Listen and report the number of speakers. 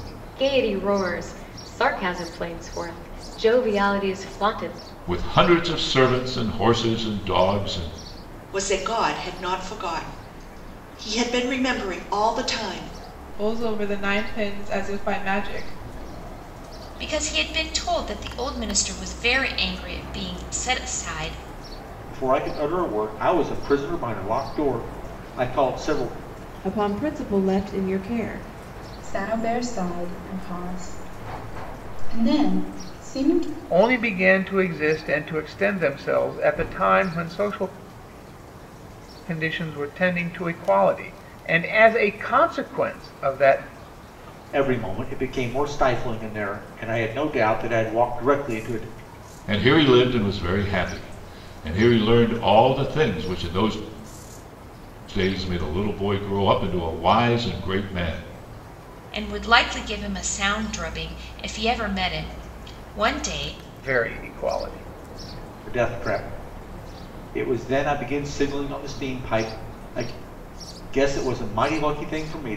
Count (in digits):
9